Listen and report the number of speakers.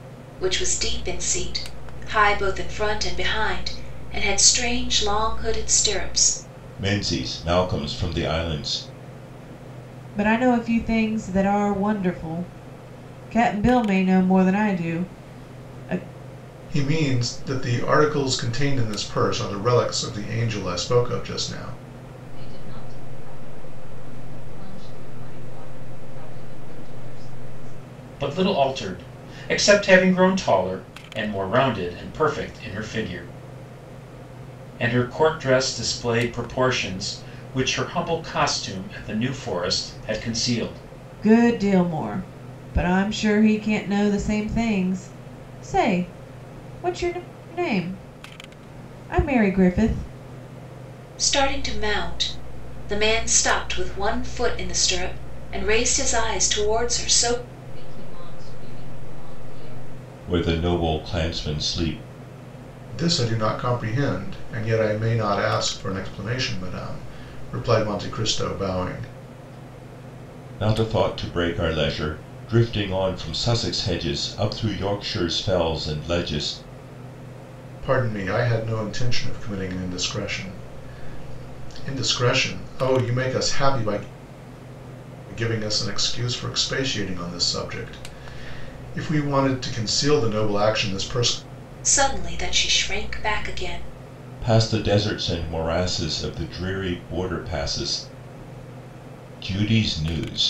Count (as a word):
six